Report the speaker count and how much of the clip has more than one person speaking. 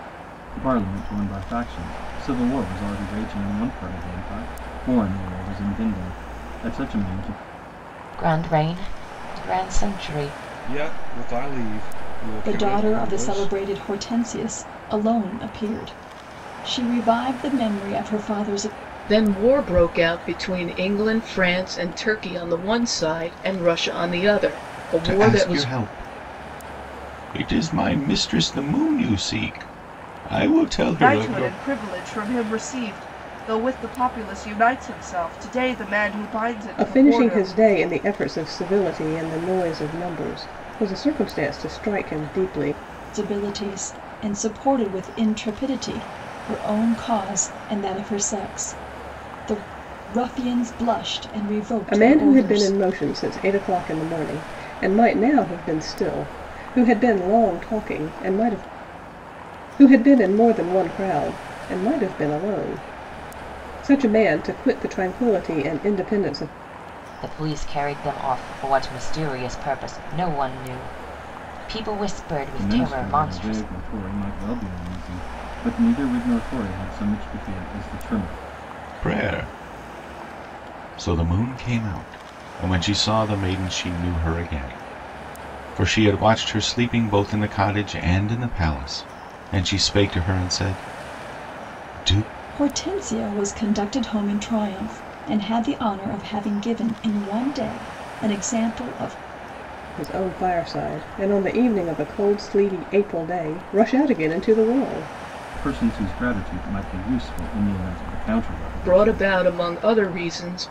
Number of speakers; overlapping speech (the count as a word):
eight, about 5%